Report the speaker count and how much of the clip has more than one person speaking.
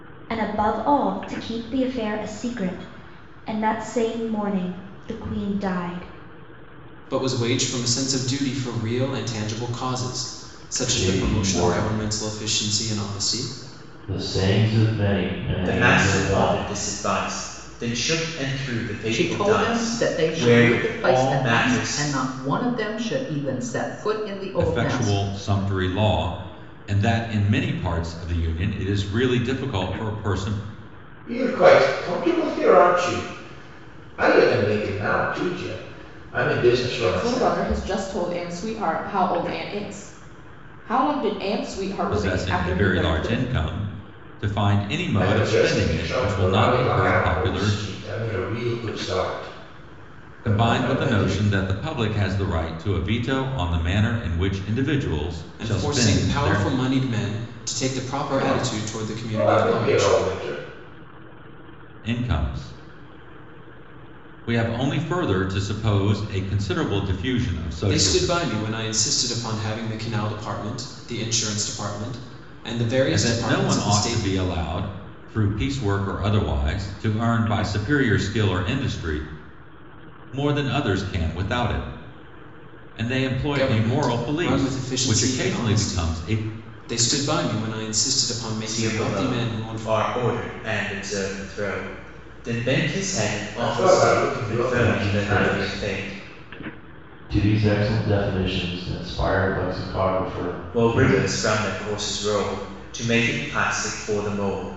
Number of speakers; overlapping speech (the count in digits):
8, about 24%